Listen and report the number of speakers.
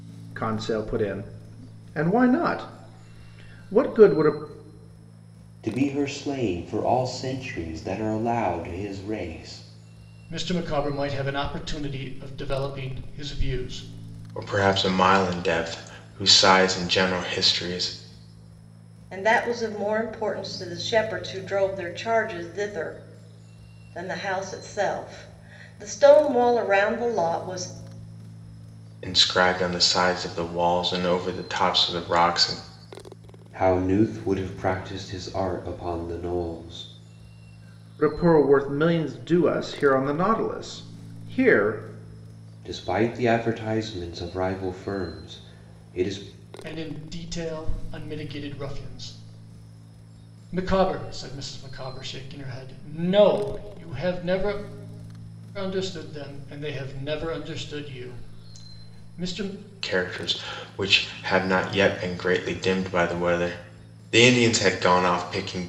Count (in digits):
5